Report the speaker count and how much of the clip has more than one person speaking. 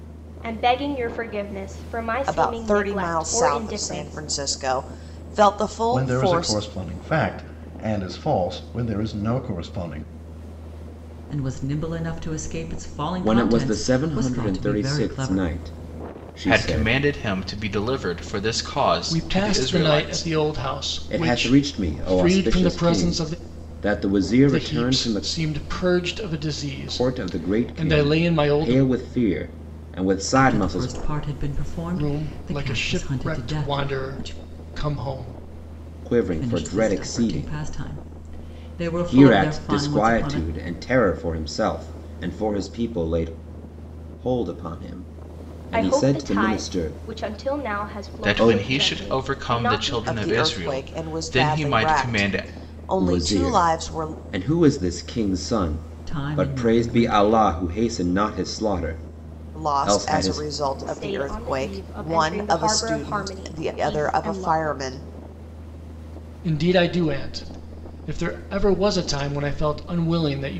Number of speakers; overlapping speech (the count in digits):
7, about 45%